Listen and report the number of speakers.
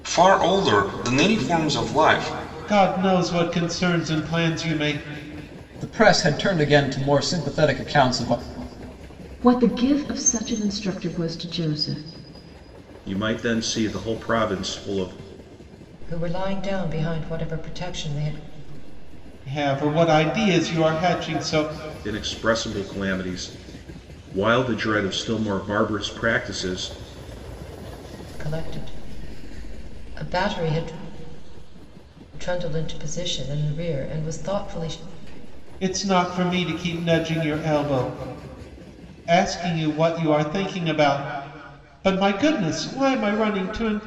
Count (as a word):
six